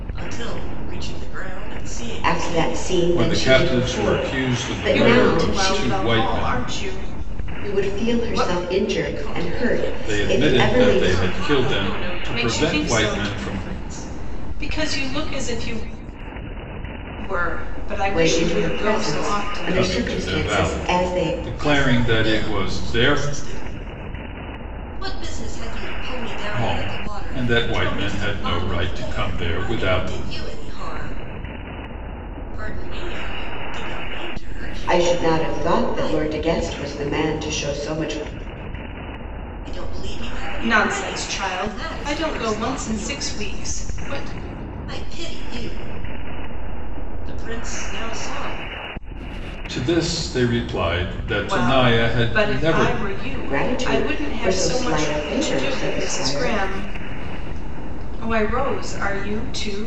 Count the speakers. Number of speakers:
four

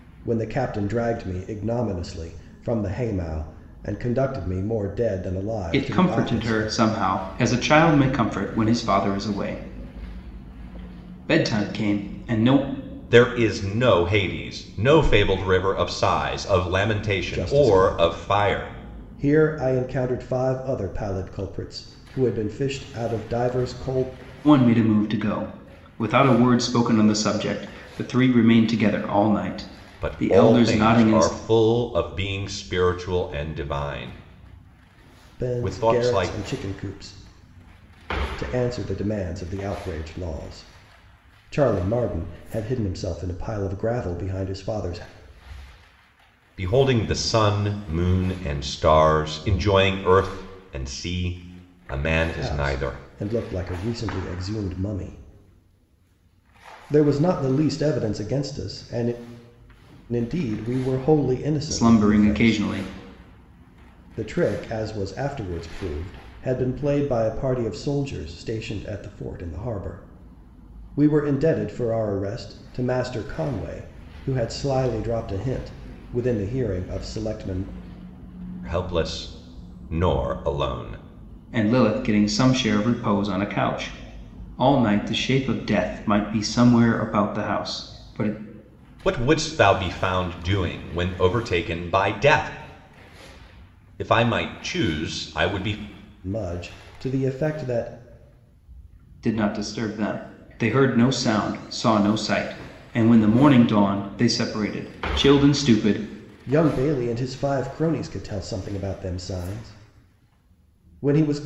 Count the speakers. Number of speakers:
three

